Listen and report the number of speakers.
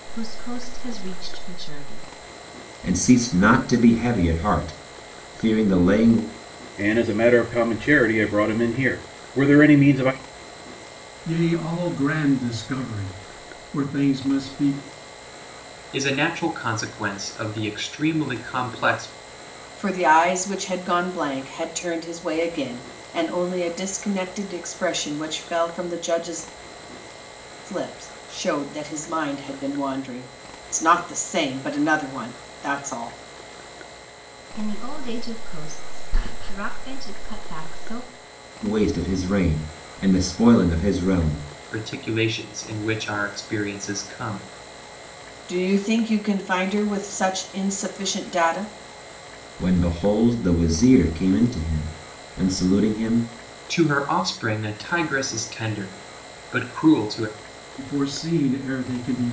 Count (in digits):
6